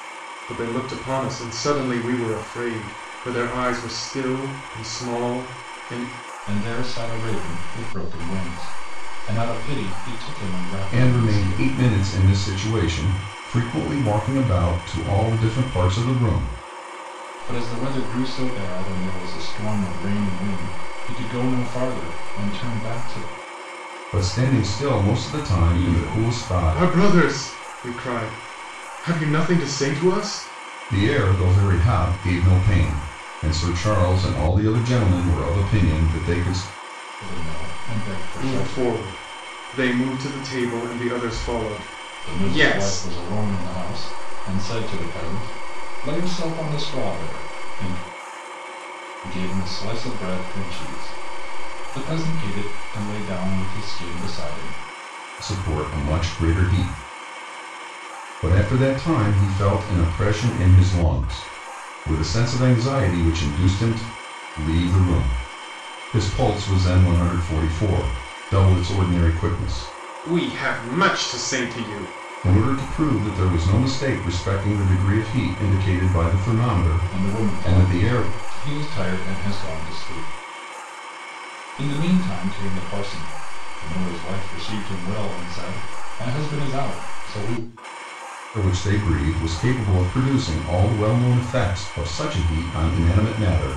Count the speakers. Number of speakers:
3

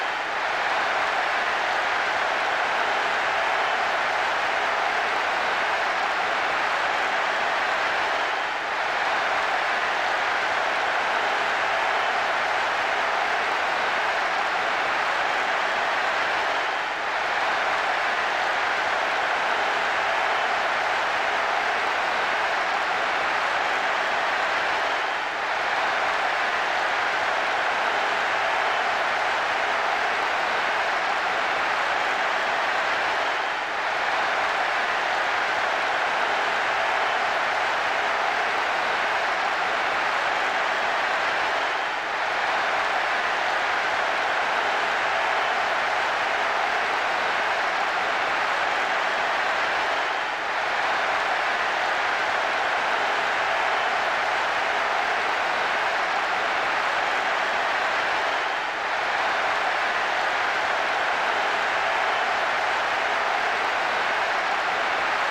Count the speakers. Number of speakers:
0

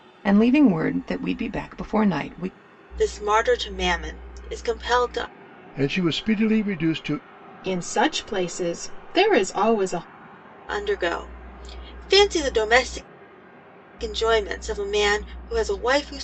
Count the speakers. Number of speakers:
4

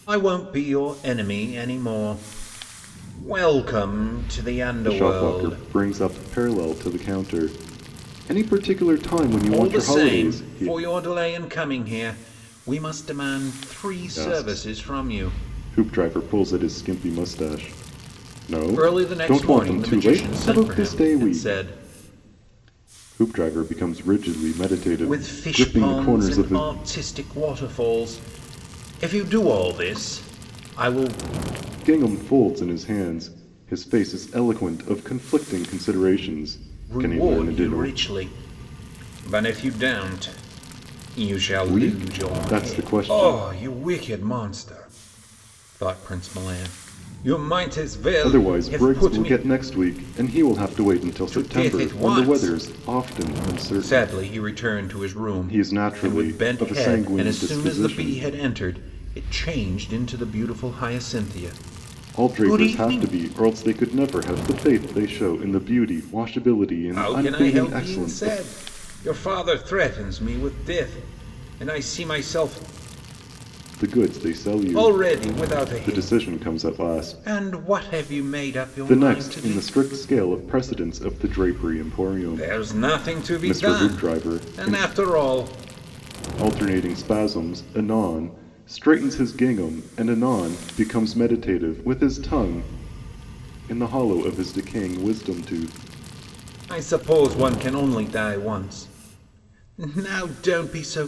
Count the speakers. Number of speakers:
2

